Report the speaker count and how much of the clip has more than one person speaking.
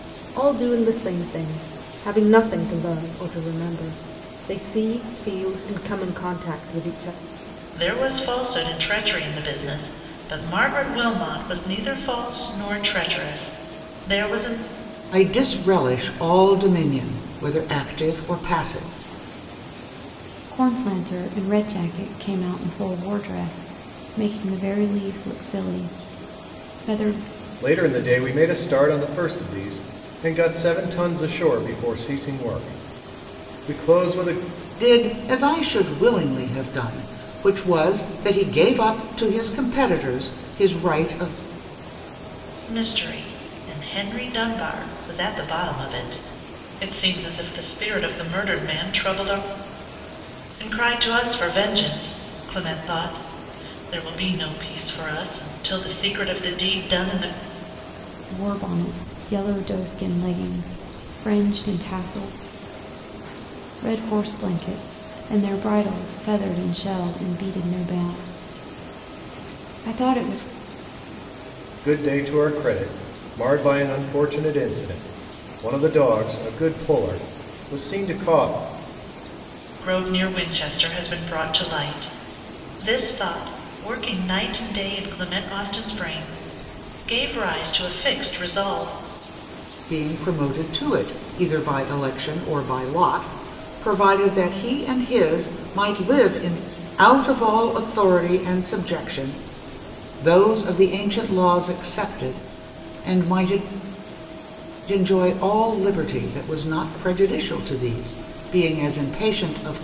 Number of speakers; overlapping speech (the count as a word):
five, no overlap